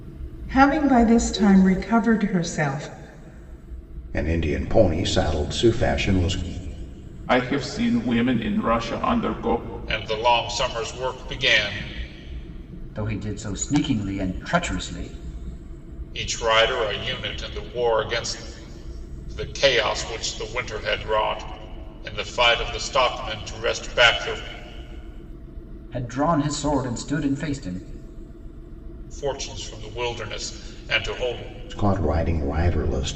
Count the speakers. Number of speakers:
5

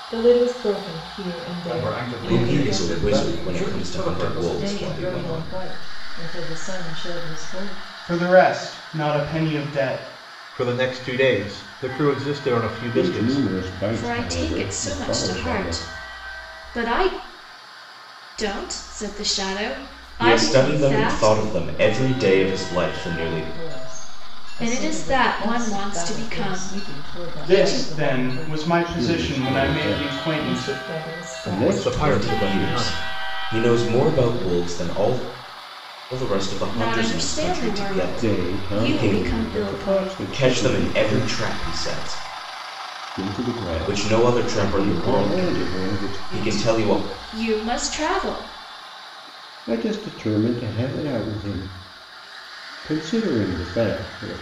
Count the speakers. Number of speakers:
8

